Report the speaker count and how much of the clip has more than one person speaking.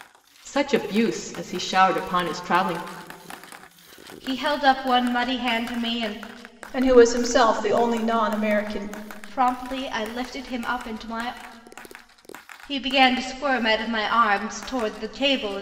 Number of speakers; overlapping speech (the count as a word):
three, no overlap